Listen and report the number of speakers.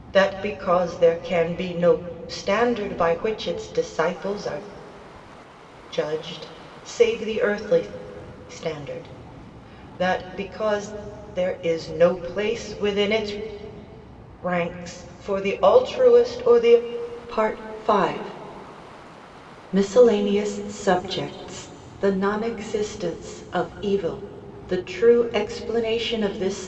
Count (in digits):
1